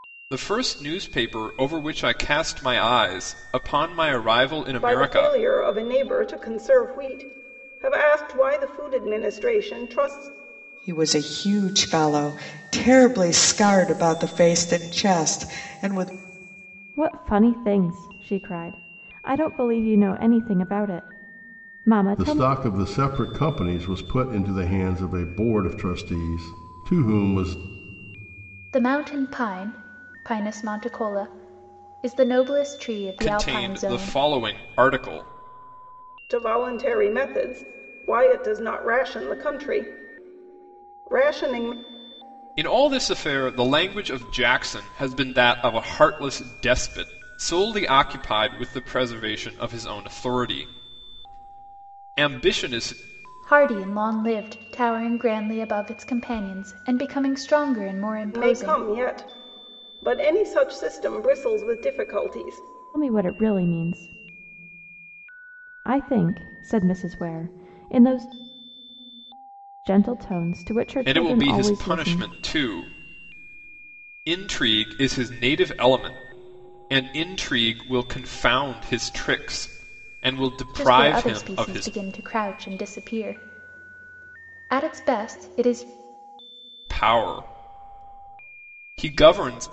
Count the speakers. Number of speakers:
6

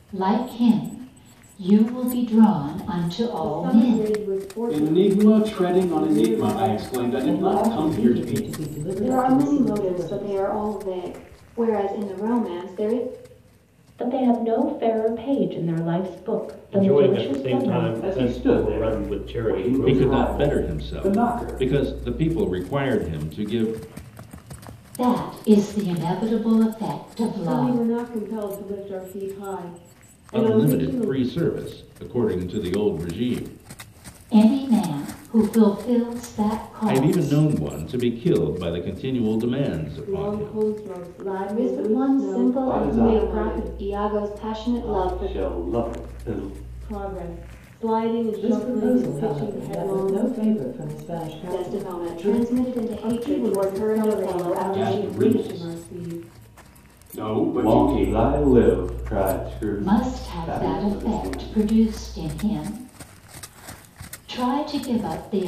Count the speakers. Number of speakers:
9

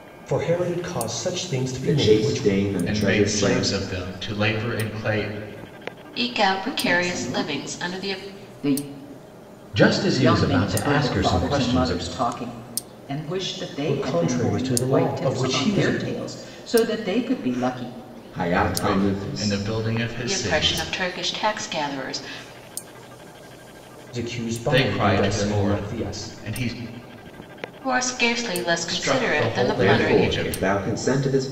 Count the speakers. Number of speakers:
6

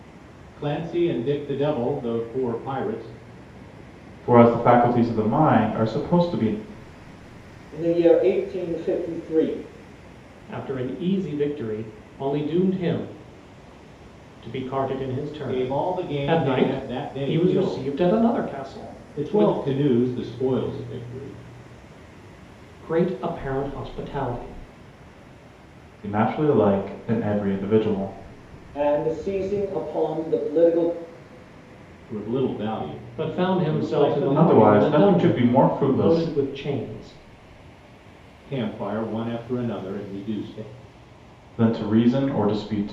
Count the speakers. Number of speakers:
4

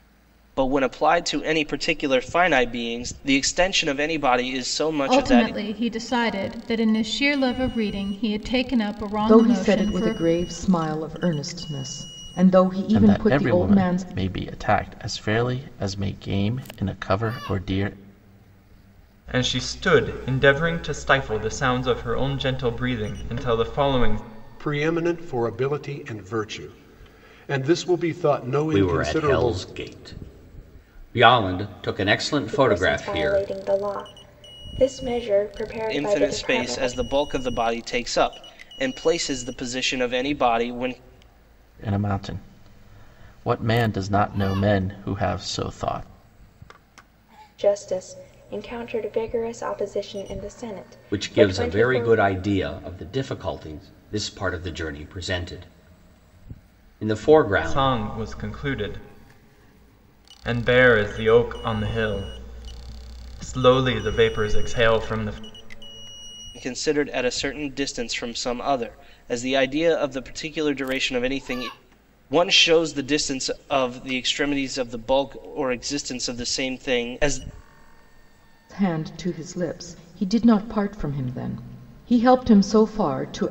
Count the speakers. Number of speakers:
8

